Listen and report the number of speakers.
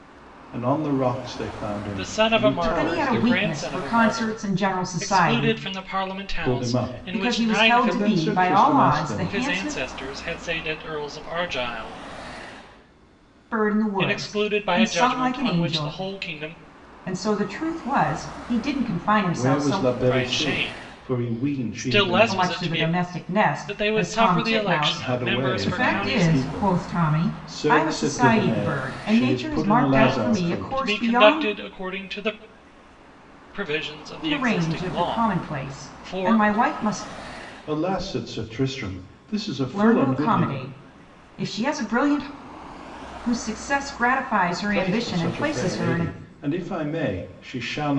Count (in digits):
3